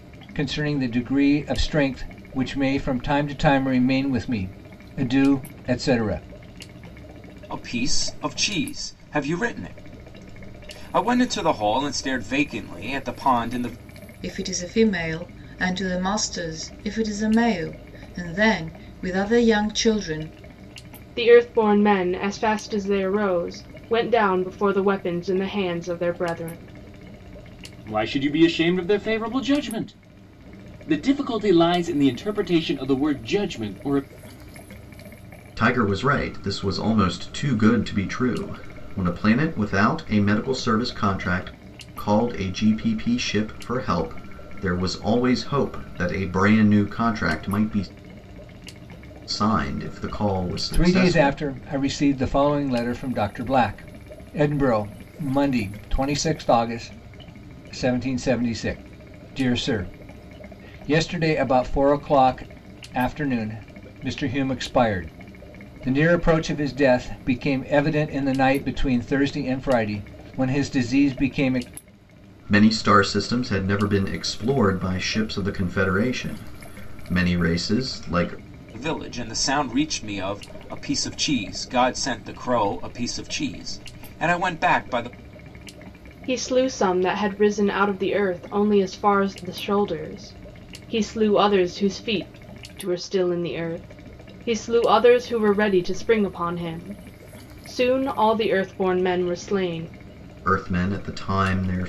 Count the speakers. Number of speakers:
six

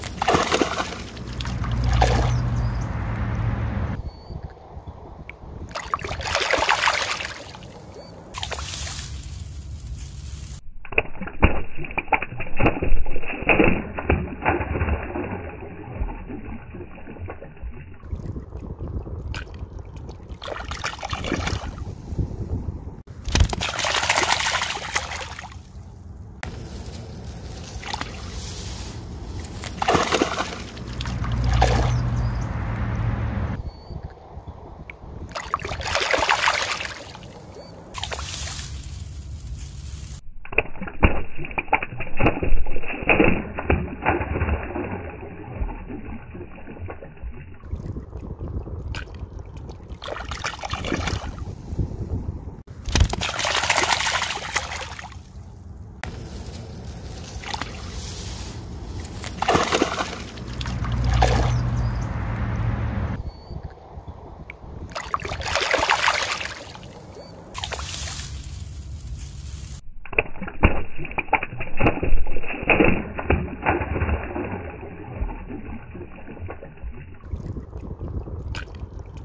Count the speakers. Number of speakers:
zero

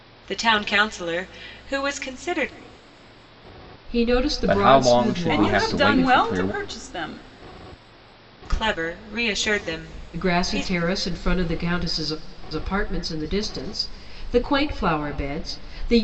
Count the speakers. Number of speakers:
four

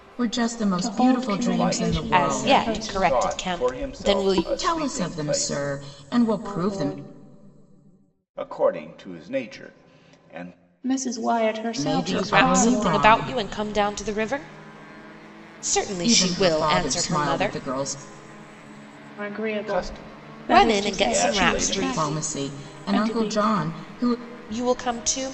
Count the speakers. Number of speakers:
four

